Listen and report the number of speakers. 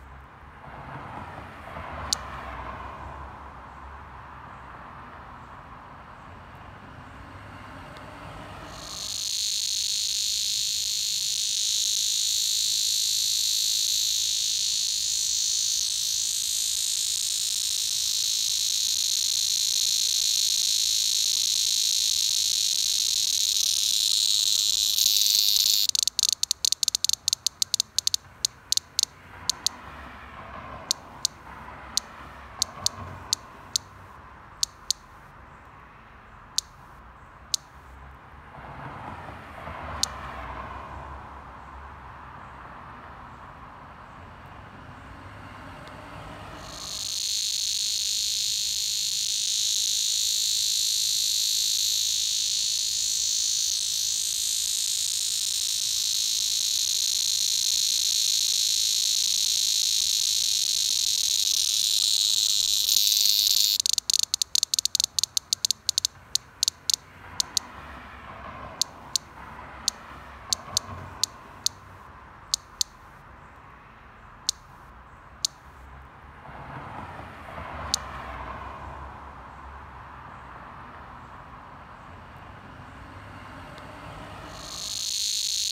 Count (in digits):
0